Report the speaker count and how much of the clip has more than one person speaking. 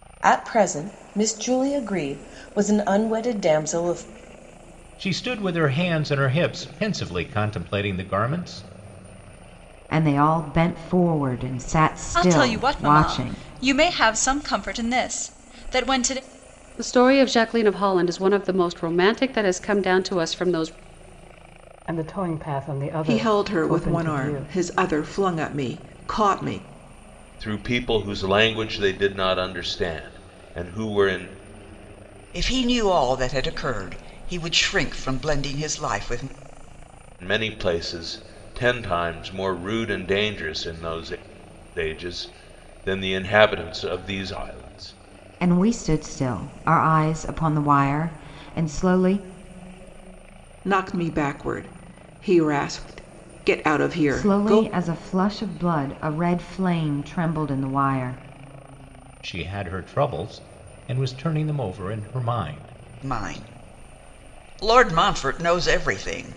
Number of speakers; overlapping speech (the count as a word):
nine, about 5%